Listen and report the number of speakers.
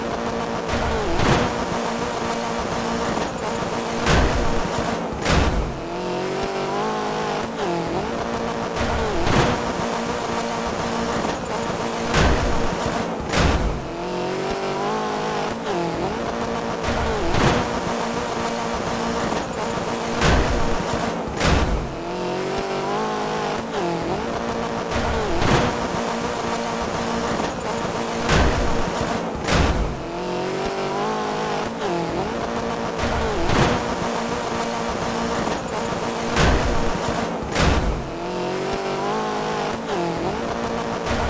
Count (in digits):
0